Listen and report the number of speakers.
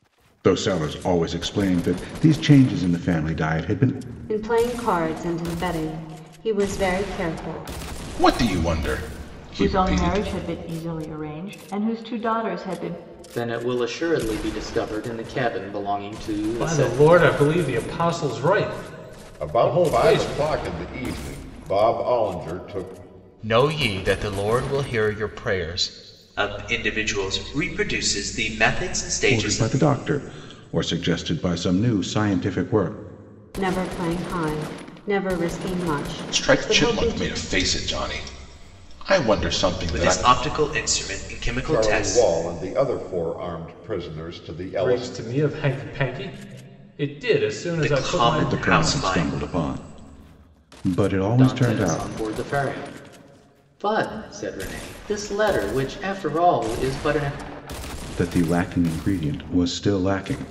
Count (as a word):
nine